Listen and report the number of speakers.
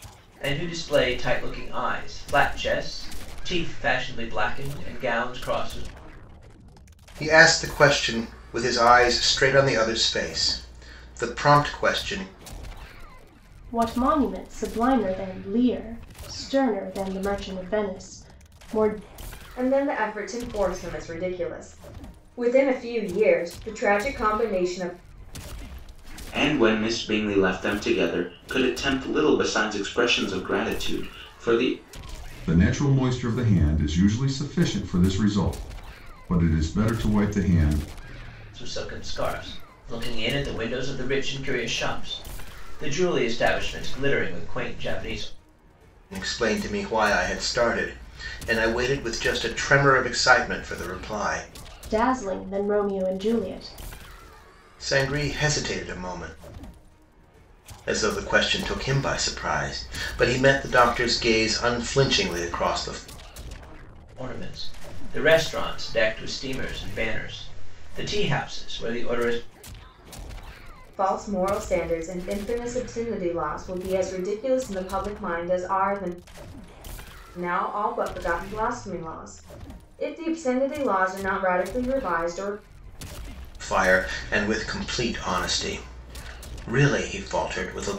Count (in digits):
6